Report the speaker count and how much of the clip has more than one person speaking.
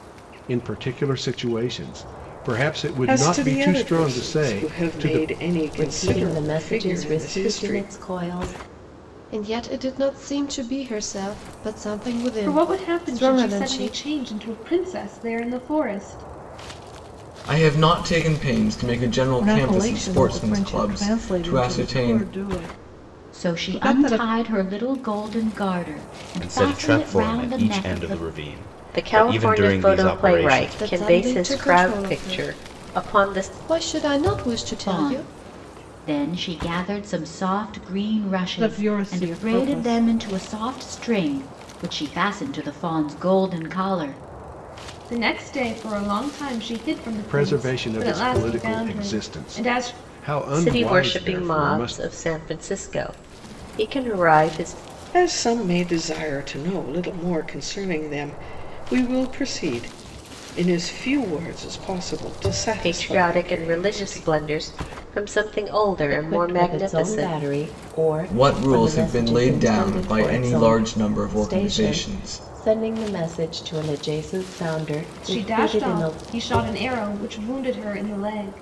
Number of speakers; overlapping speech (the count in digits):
10, about 38%